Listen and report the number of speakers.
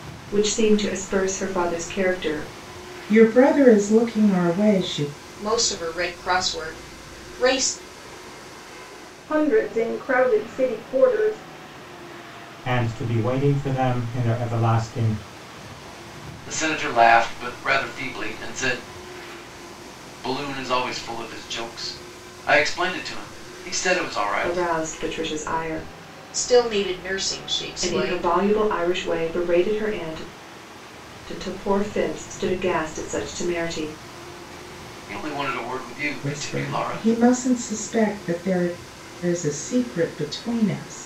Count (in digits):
6